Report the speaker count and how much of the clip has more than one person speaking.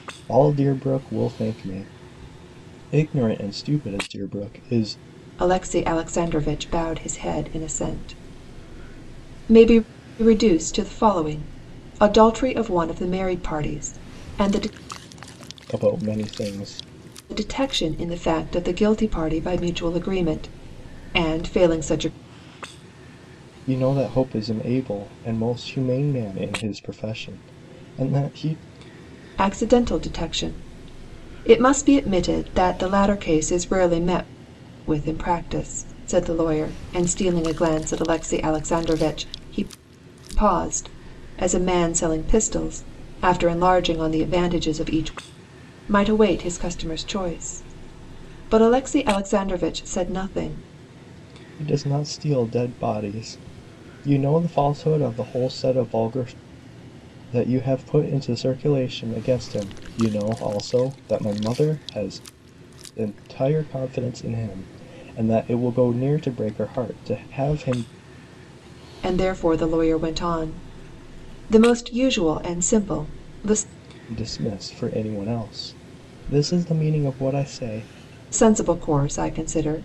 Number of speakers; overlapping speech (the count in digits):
2, no overlap